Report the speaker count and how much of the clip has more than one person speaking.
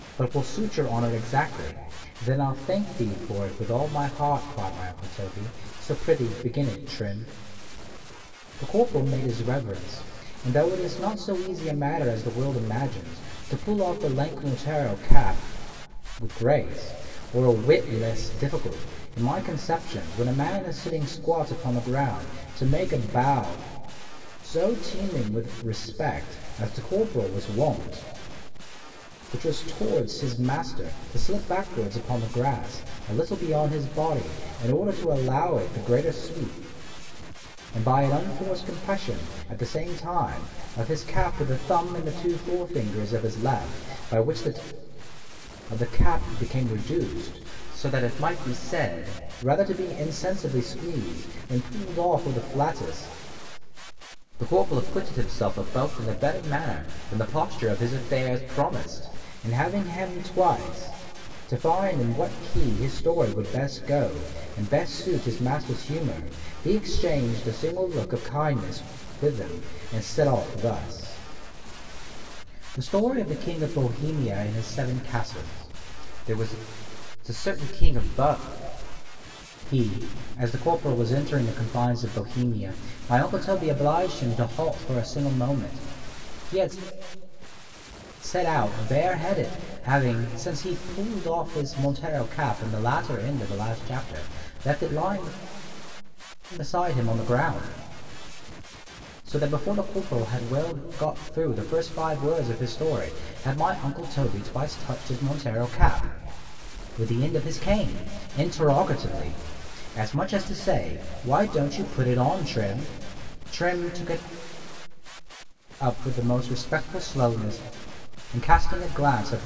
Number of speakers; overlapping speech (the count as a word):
one, no overlap